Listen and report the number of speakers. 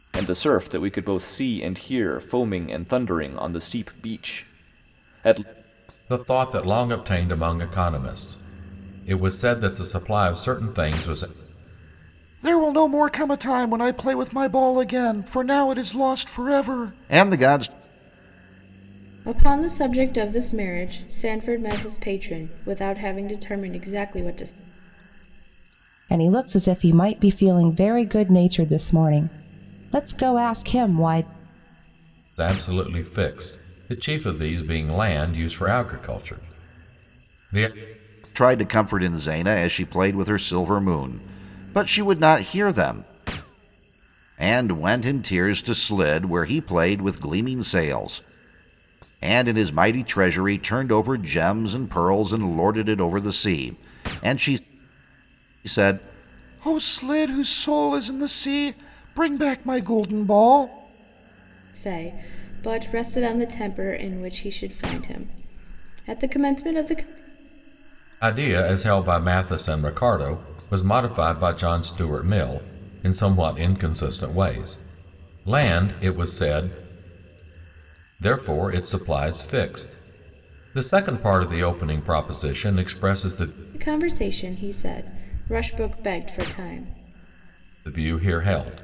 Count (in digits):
5